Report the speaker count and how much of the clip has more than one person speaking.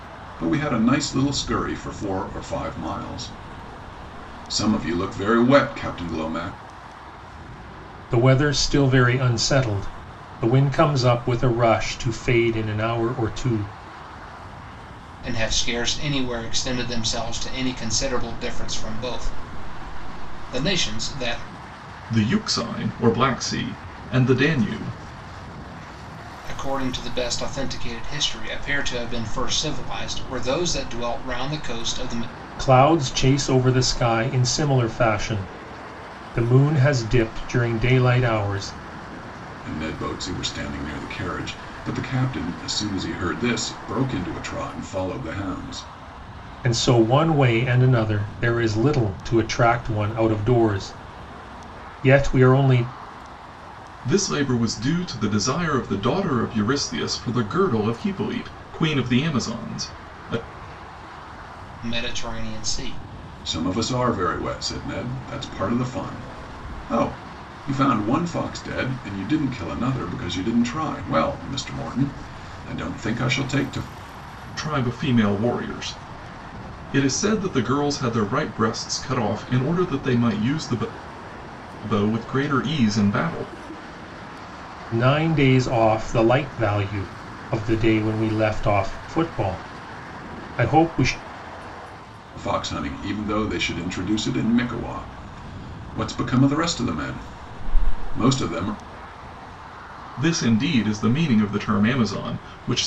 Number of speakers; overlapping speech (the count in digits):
4, no overlap